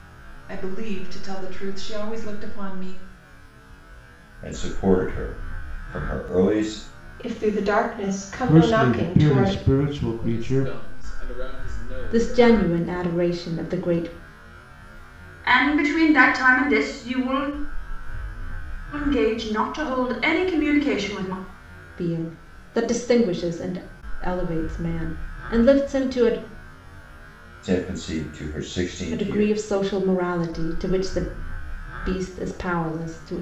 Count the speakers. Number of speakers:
seven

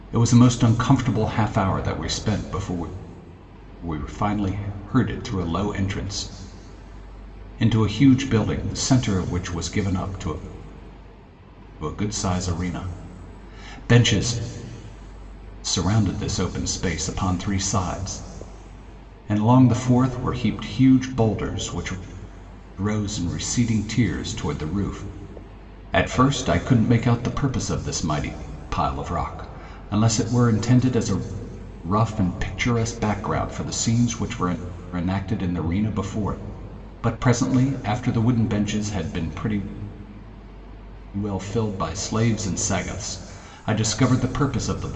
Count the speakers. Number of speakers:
one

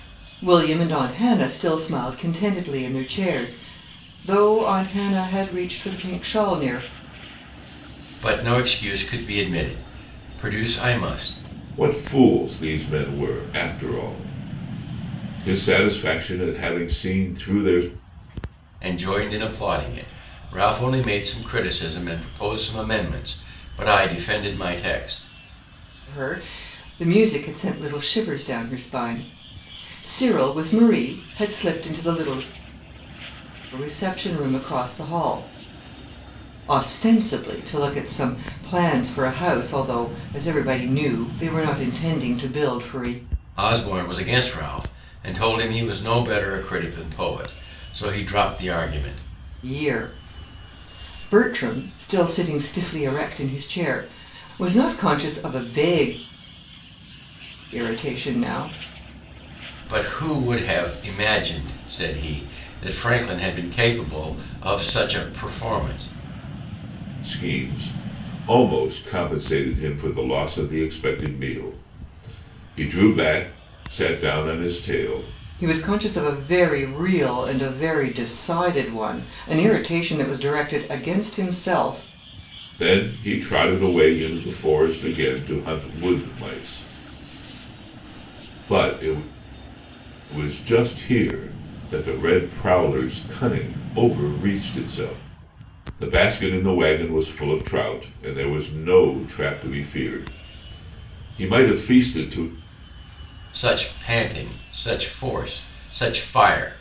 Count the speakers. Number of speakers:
three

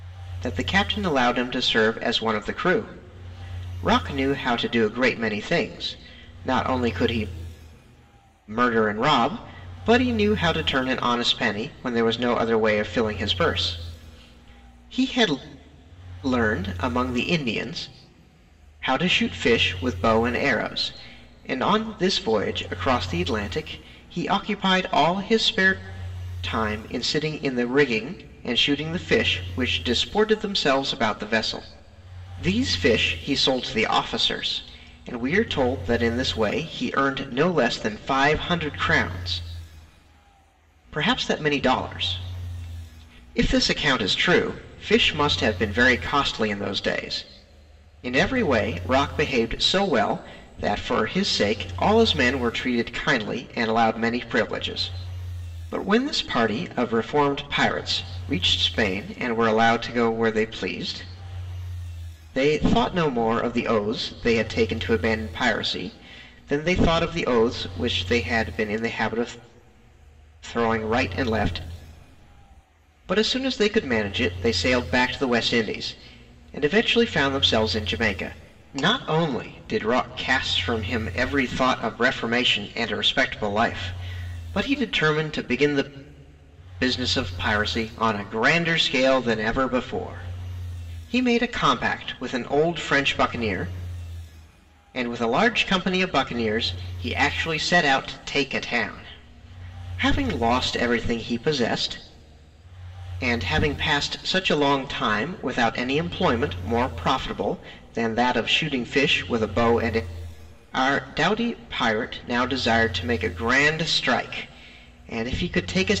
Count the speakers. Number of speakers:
one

